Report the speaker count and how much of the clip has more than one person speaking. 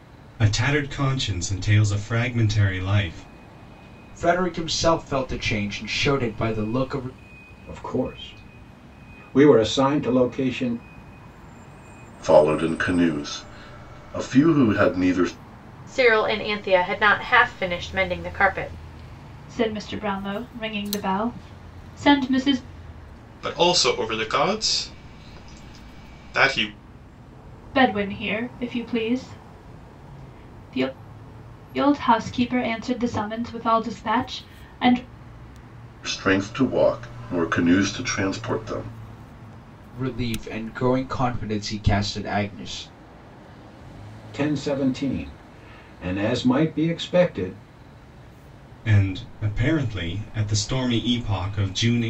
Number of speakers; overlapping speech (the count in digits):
7, no overlap